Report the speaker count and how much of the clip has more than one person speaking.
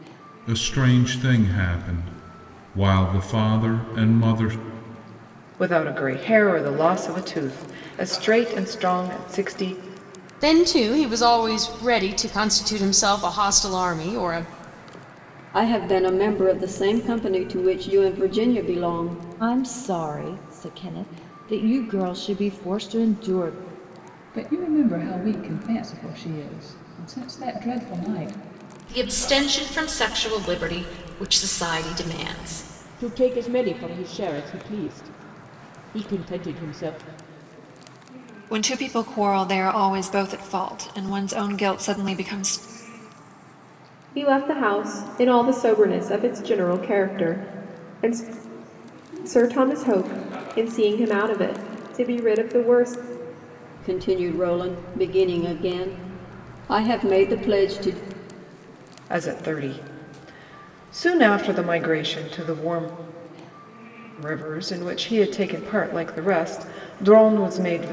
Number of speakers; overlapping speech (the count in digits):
10, no overlap